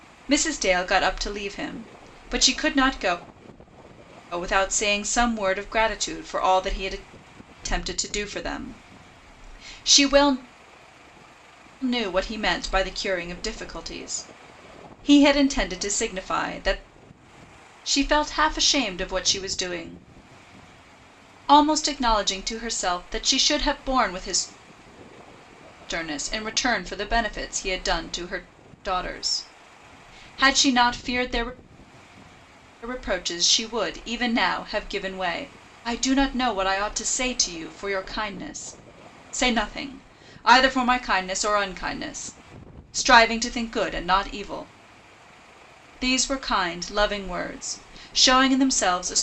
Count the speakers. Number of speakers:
1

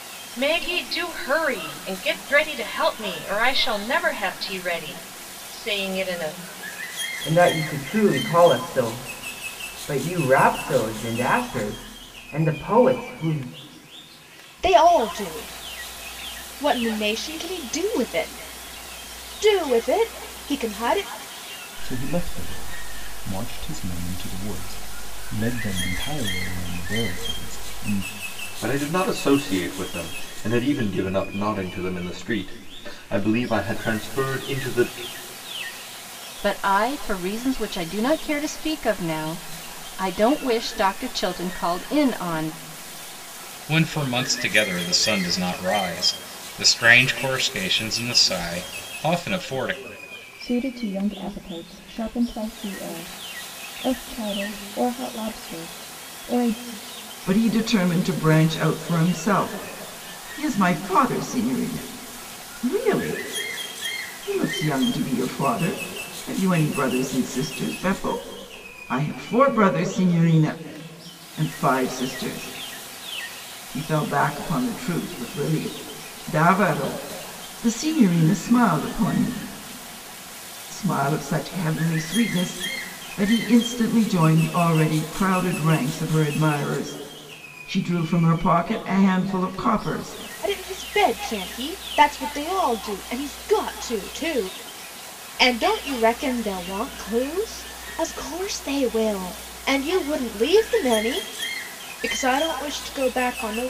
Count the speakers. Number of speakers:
9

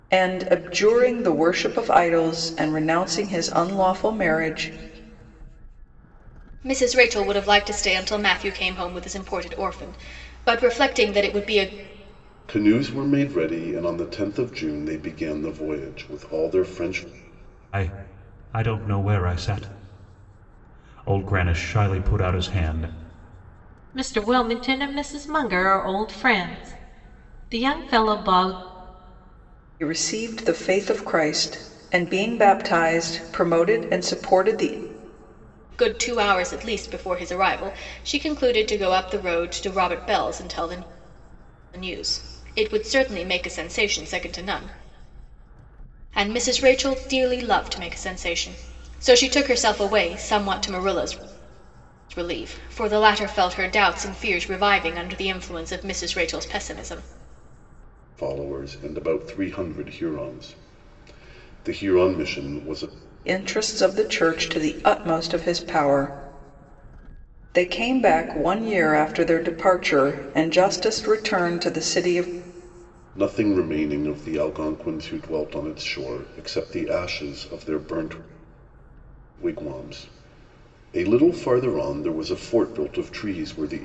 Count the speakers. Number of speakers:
5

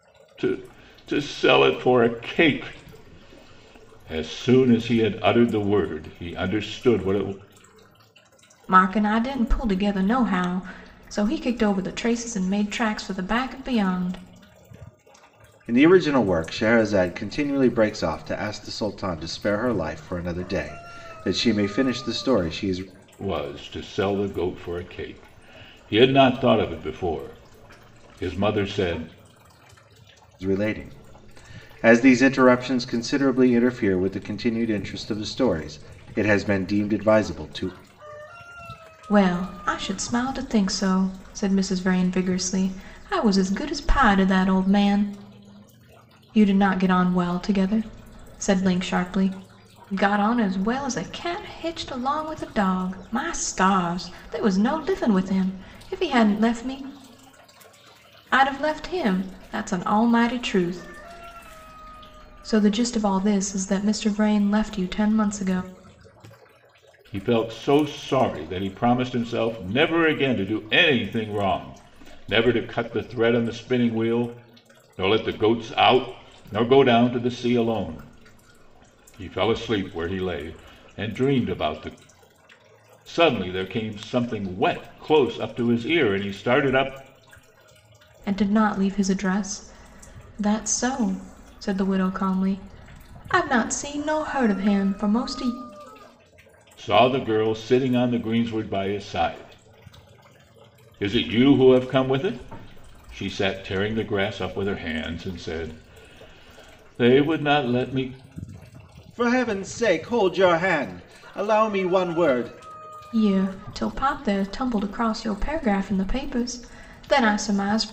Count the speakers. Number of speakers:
3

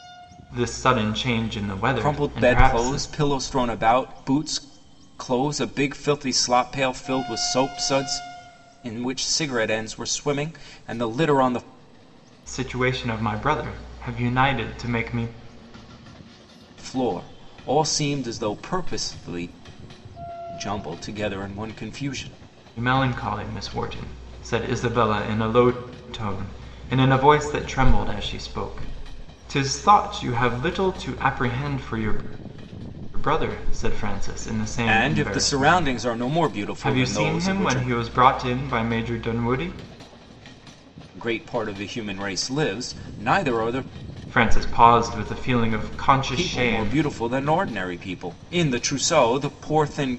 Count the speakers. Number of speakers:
2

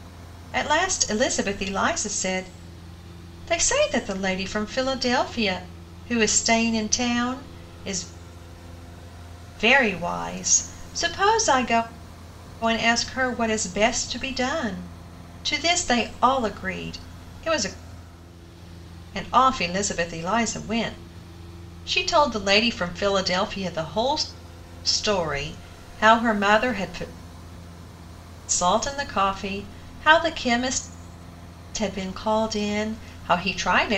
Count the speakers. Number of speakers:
1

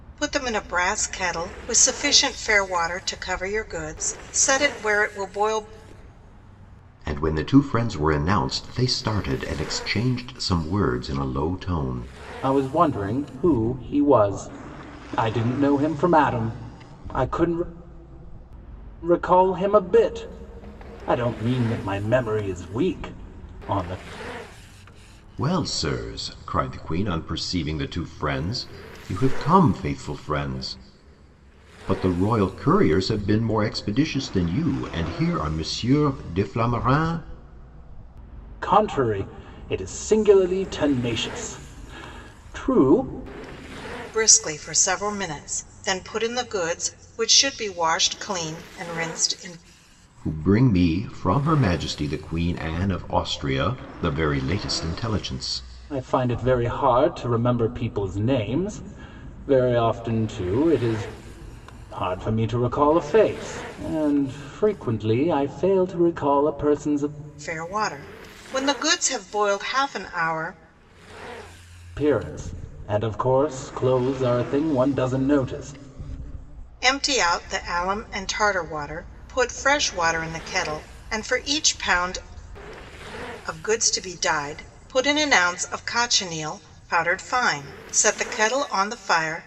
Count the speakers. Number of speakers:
3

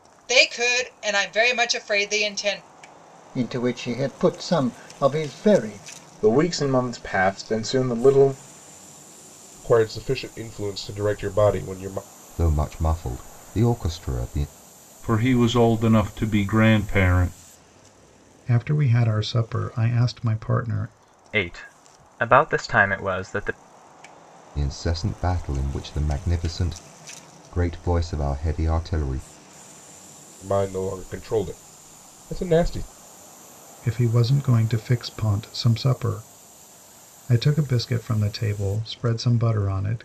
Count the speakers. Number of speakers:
8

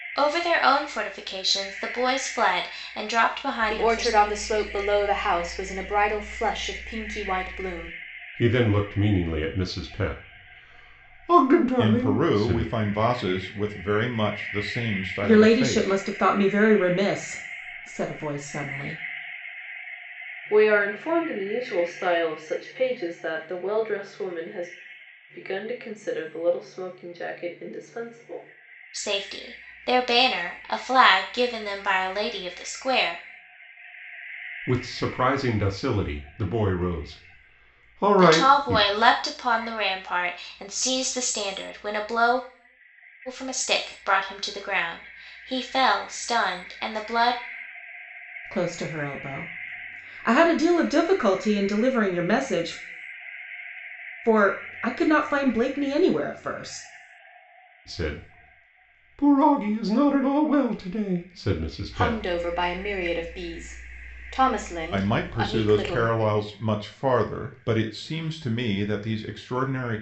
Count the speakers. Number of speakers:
6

